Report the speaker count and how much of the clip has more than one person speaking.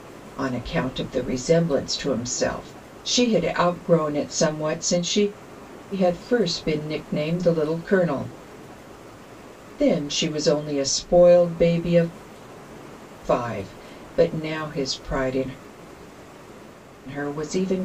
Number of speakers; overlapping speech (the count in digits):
1, no overlap